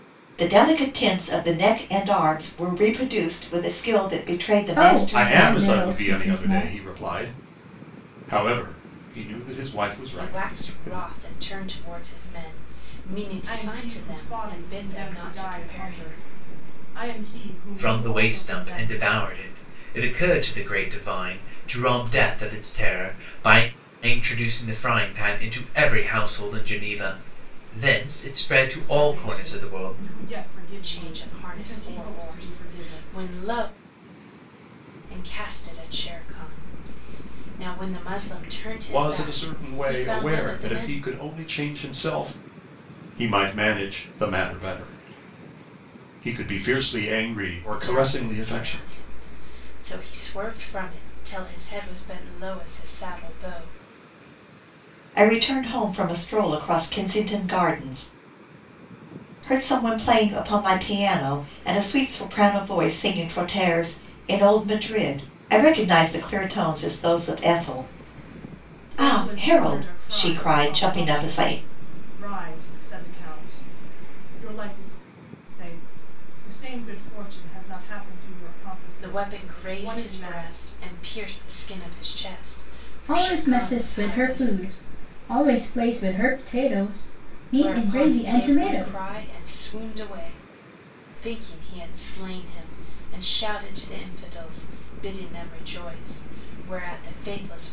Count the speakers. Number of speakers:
6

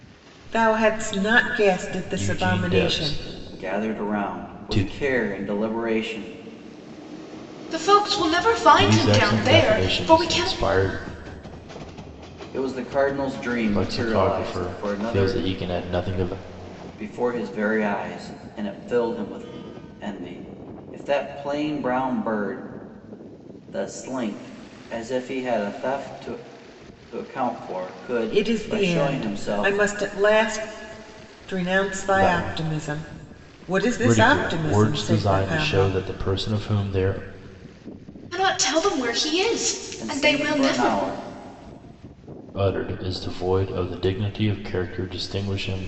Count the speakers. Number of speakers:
4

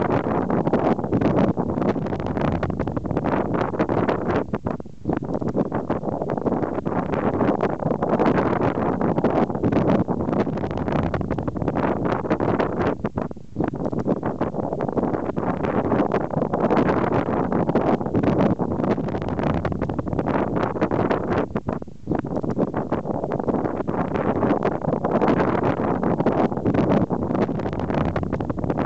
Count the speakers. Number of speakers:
0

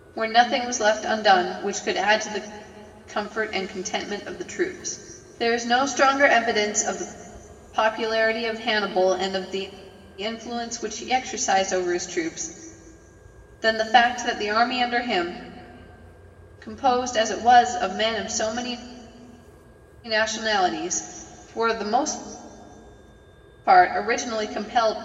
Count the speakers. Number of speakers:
1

